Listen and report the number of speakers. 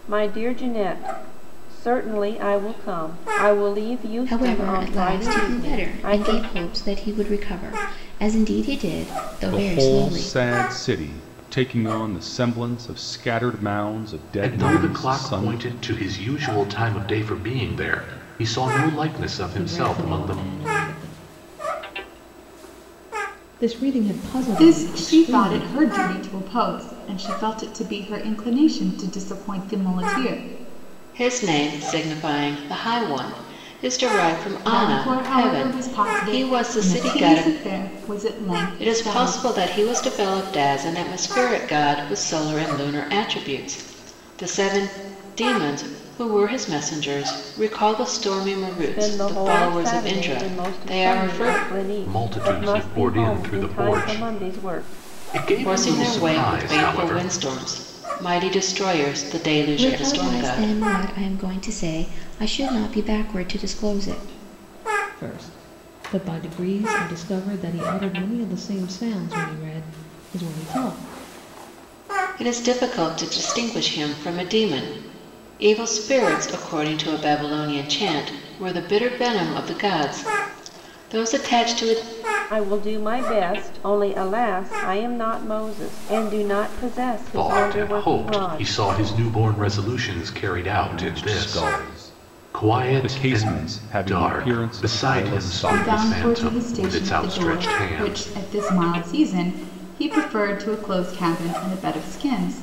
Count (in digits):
7